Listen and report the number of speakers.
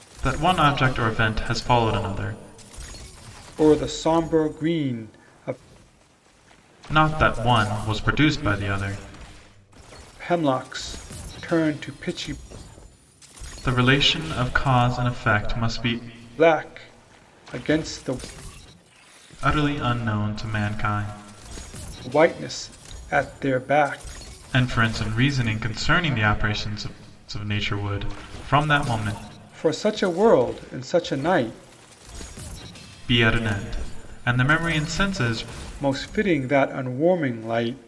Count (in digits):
2